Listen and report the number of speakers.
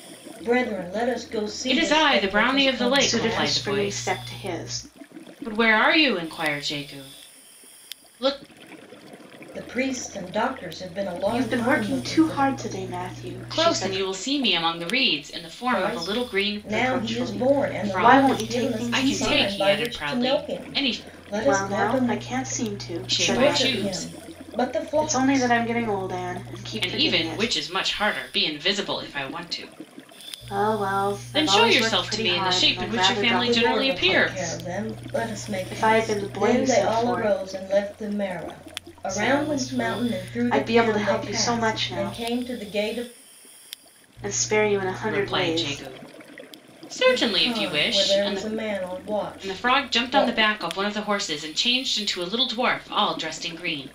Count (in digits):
3